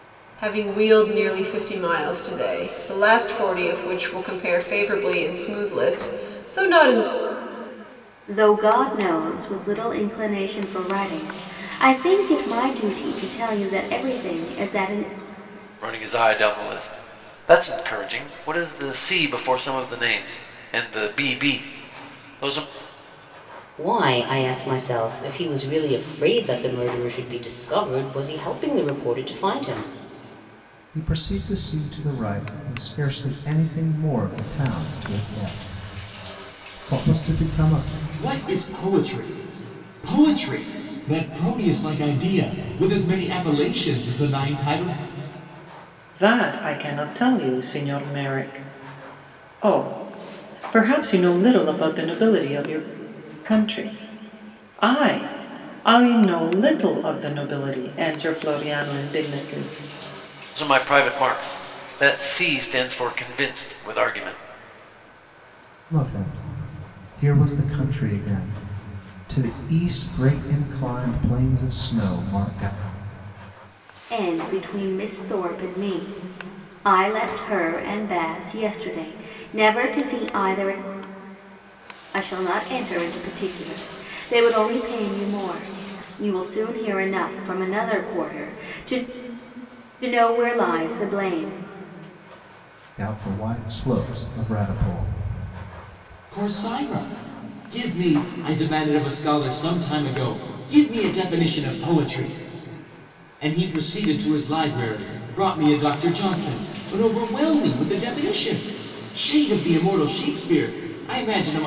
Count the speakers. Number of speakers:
seven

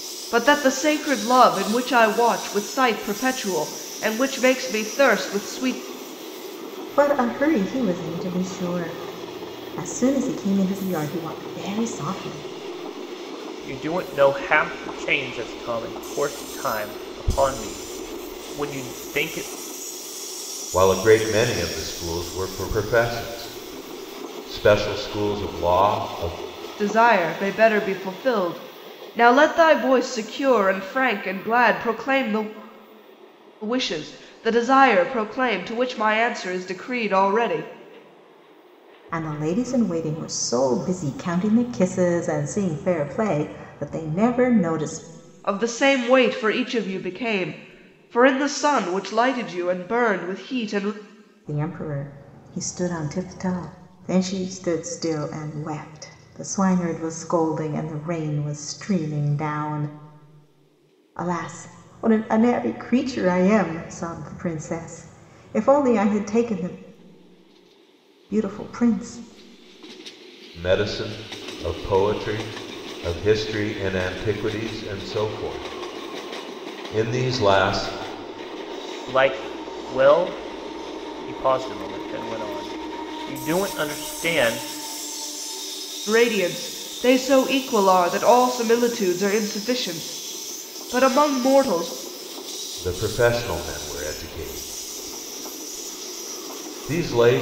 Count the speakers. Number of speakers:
four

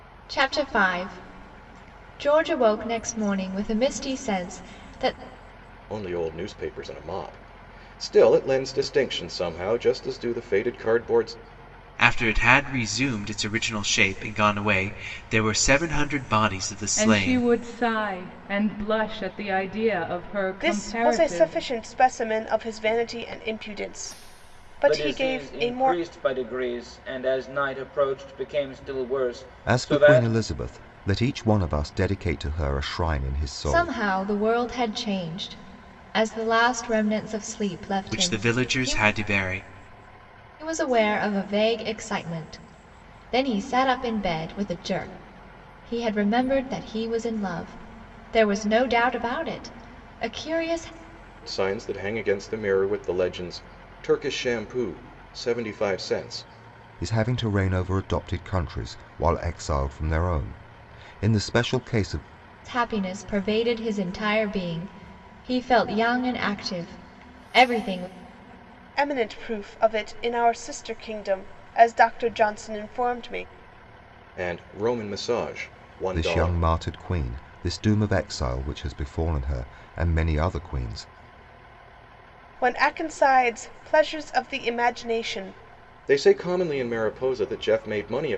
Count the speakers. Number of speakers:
seven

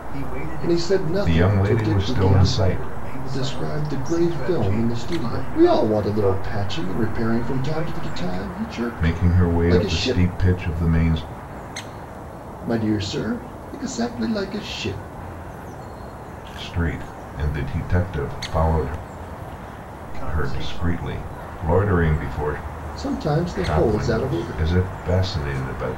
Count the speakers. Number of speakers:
three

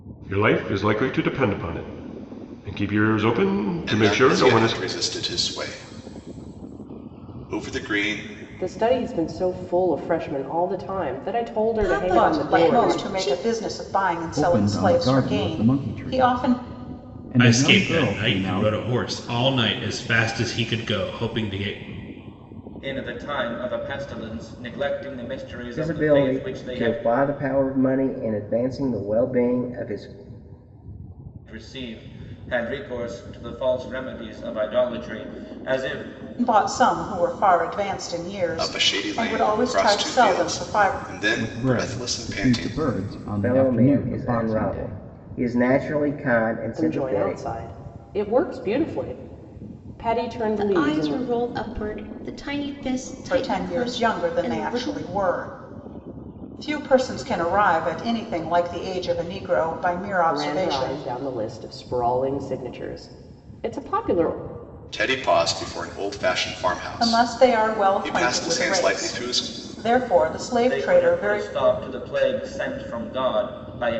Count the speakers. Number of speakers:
nine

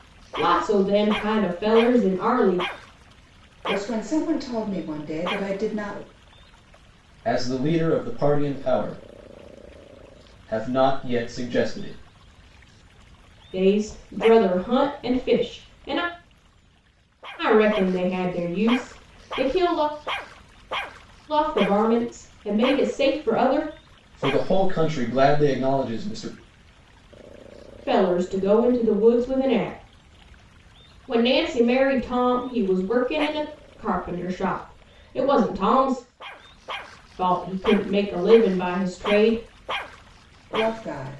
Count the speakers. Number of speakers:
three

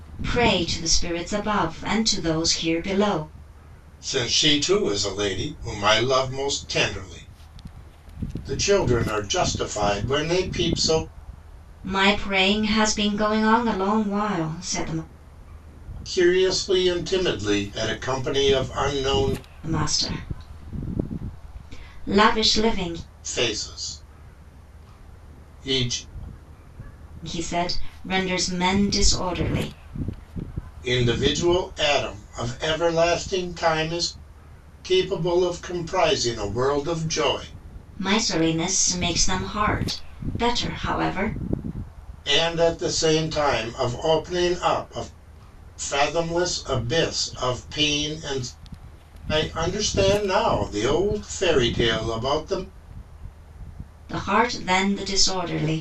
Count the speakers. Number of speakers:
two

